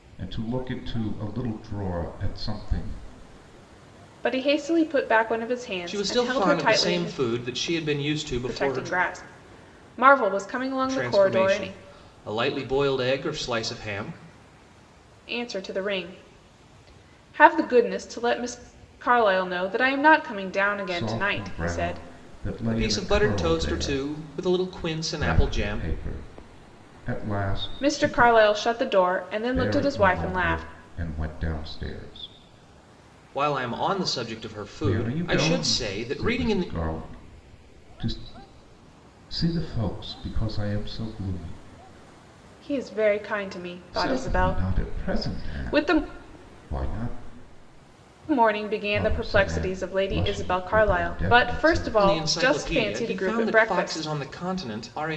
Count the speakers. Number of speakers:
three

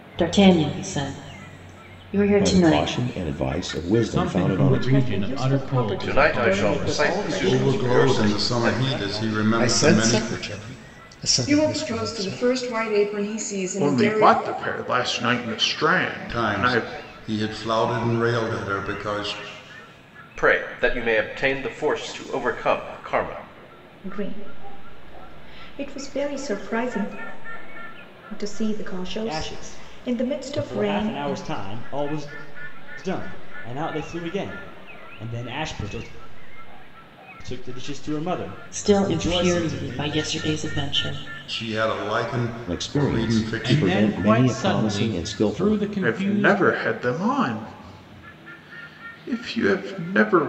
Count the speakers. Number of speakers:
ten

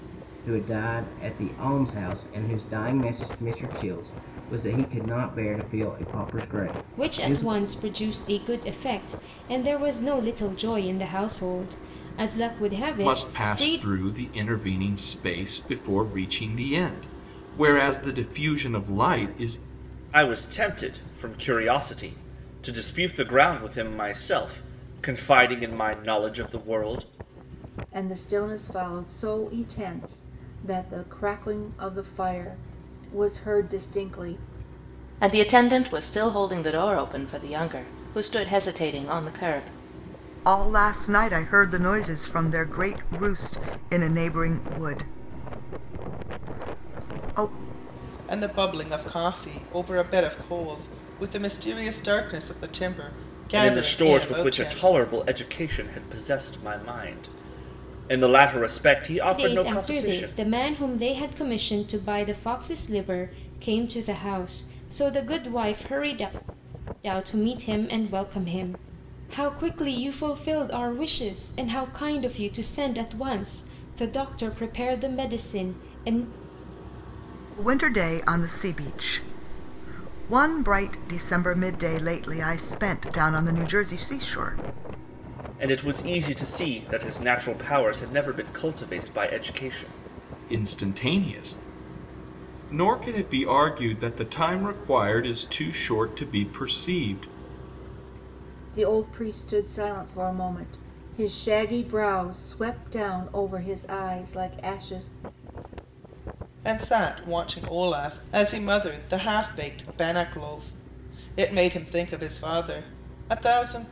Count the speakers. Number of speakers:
eight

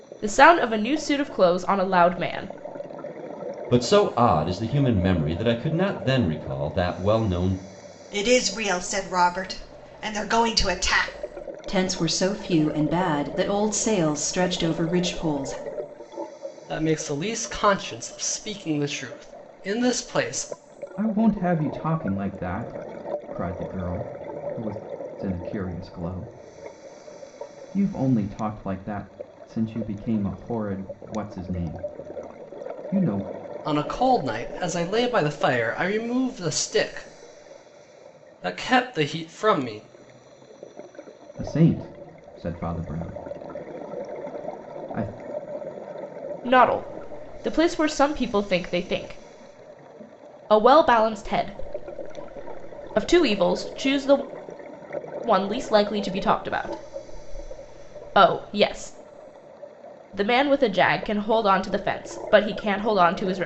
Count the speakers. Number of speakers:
six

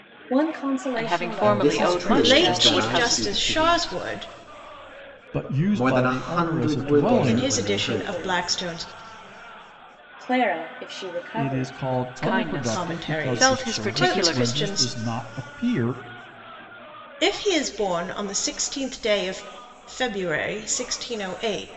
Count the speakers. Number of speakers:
five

